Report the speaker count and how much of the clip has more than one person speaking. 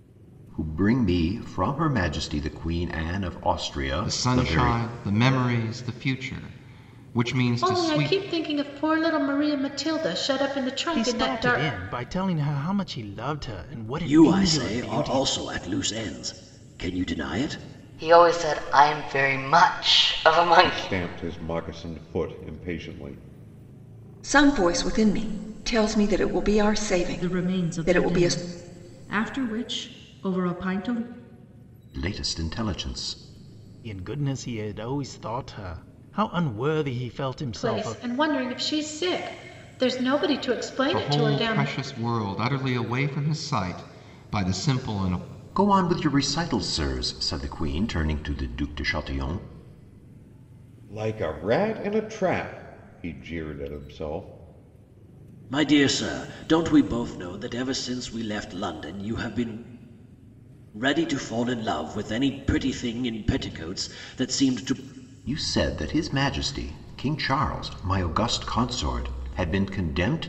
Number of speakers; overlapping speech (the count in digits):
9, about 10%